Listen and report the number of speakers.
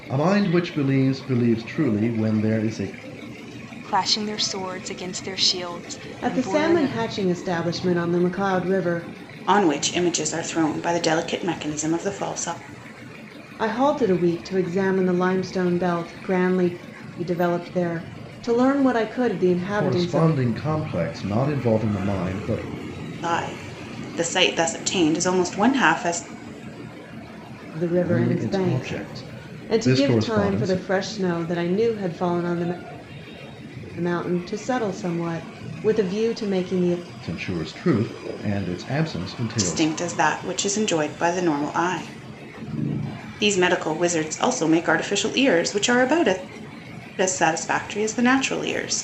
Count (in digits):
4